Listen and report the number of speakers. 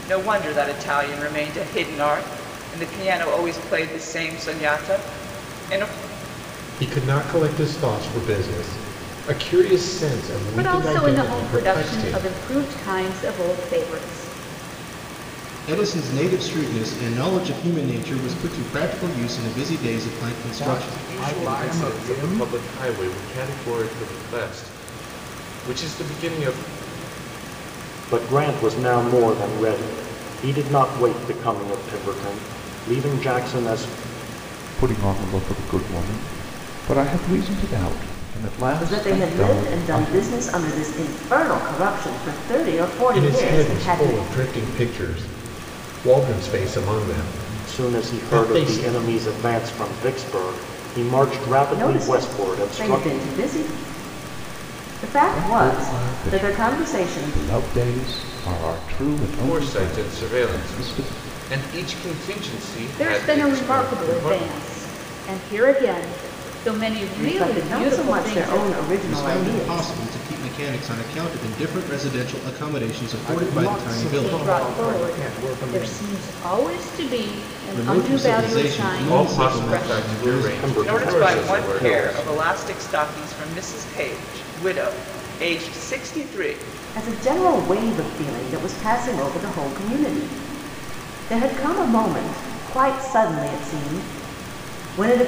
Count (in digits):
9